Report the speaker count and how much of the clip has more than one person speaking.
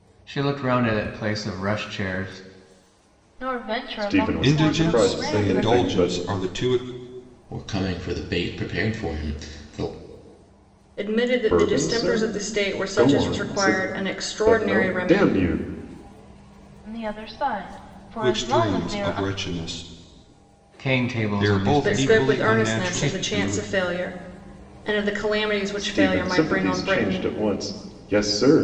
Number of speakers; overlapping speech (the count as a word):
six, about 37%